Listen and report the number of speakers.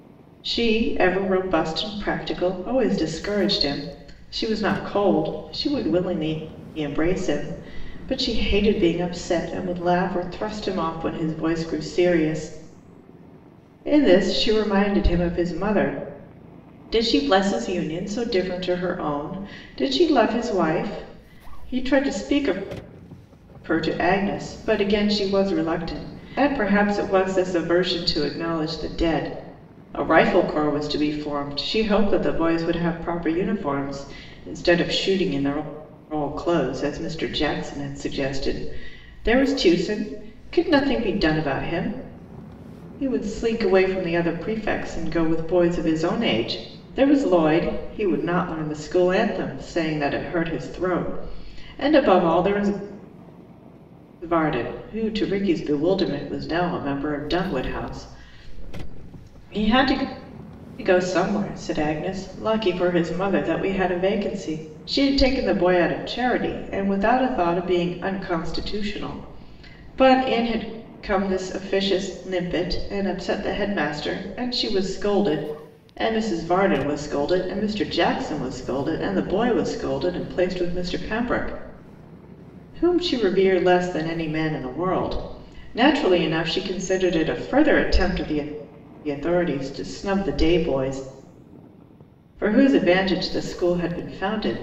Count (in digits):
1